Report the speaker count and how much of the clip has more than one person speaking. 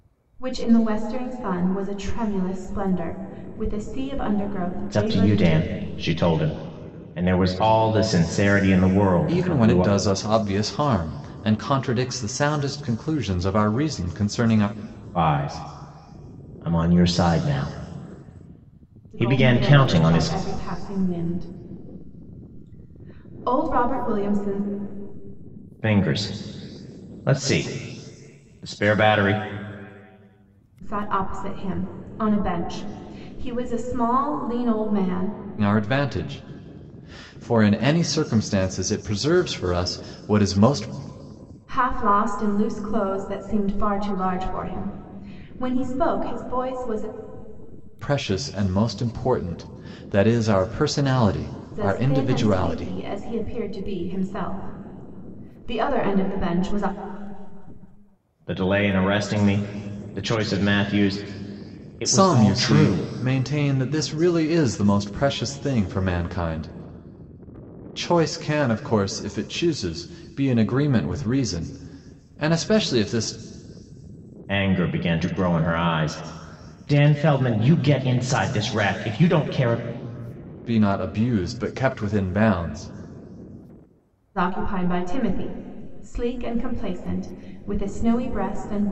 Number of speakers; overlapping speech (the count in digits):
3, about 6%